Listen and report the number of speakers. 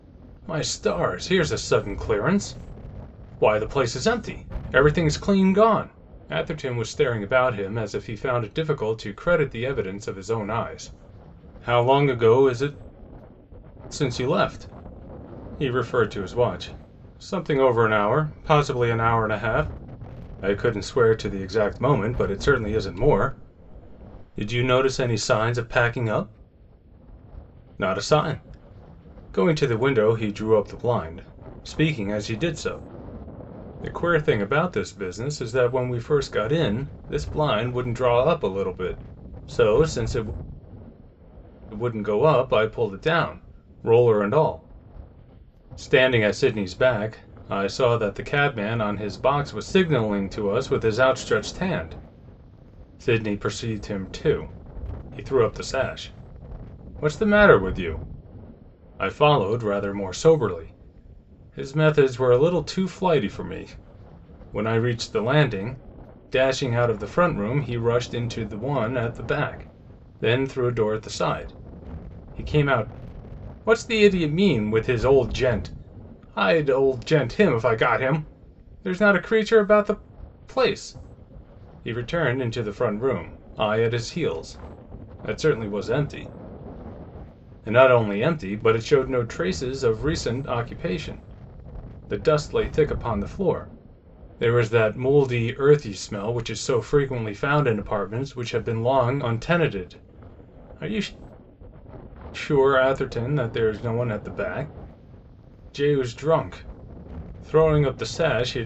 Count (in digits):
1